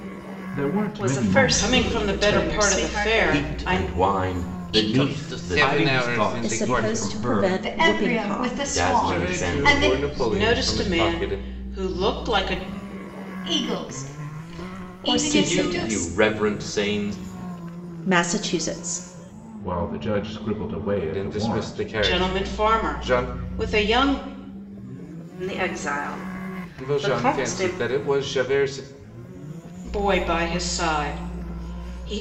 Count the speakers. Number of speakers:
8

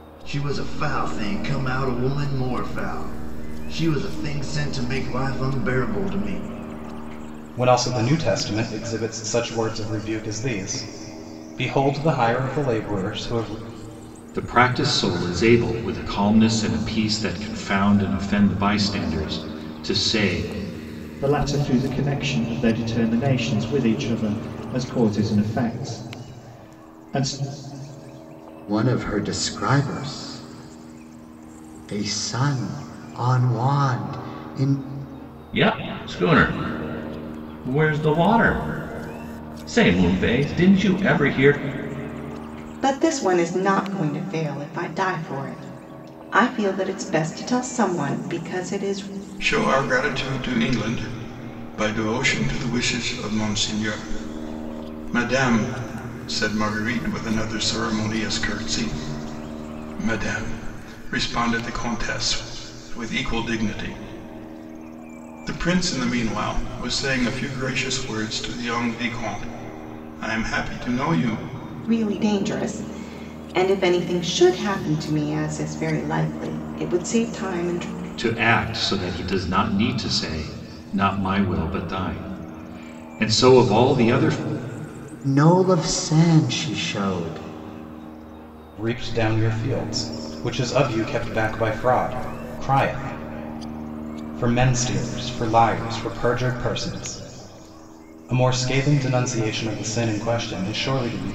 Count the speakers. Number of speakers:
8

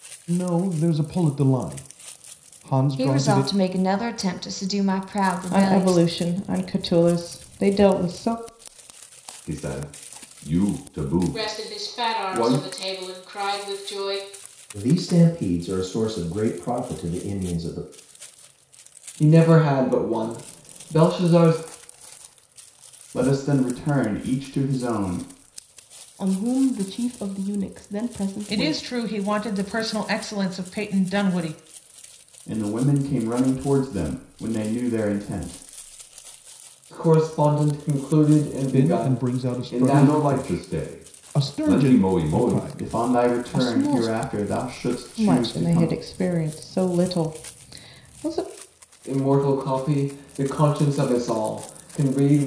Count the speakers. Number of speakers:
10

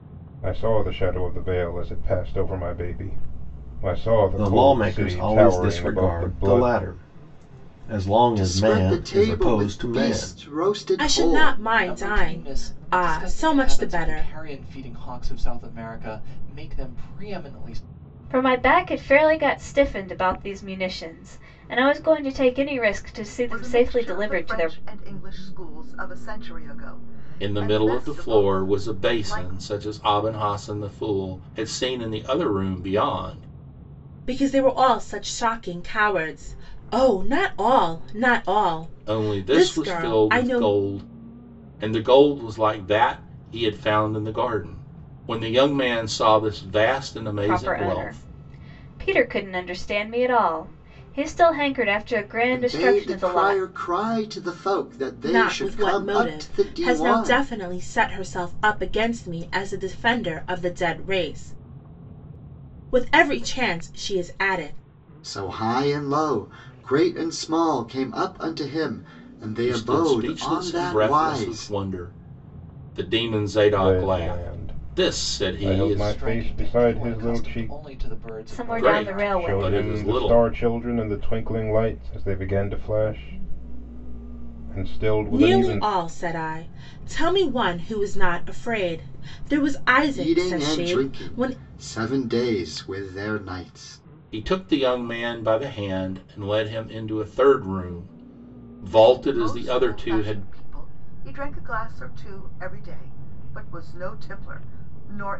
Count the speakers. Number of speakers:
8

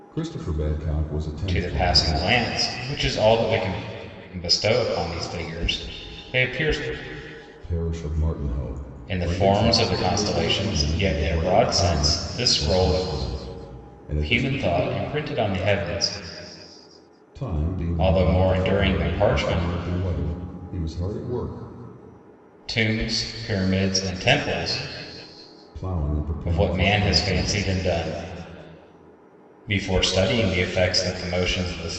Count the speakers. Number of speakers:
2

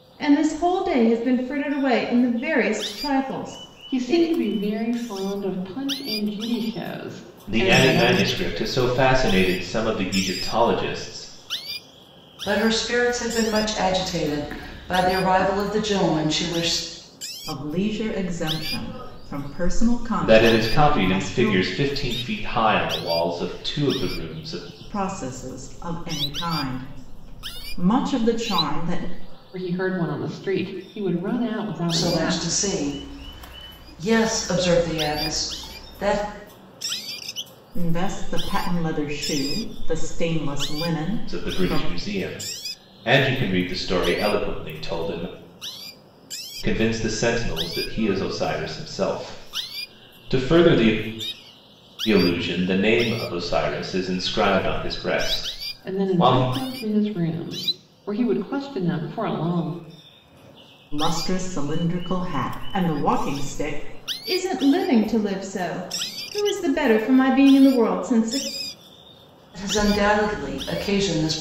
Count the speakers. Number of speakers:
5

